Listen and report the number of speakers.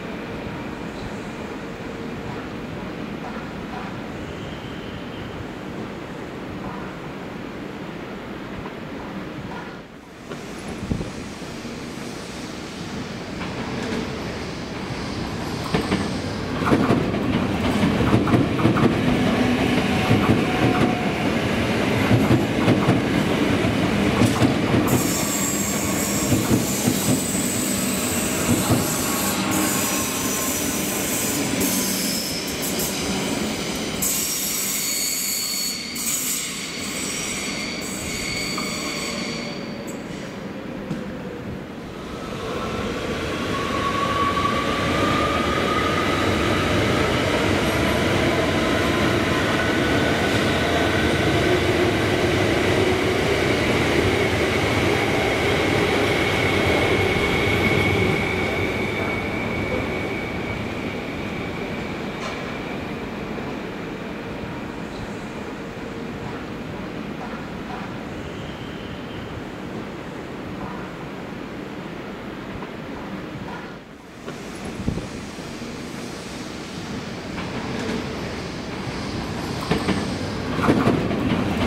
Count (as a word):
zero